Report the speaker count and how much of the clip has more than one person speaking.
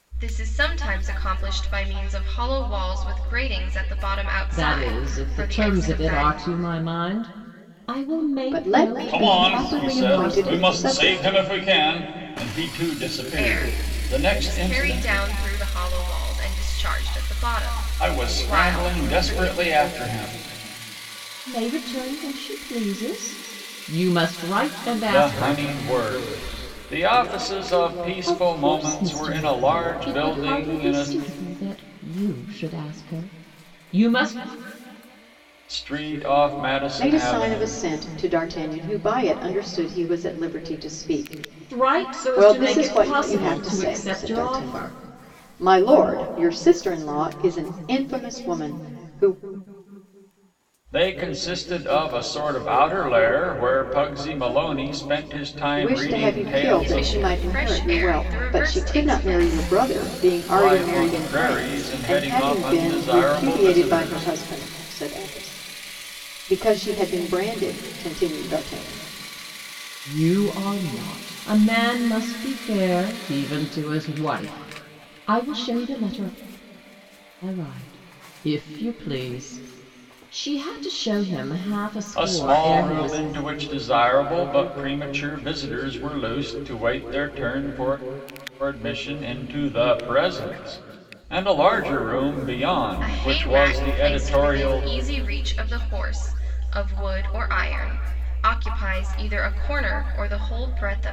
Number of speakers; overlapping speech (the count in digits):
4, about 26%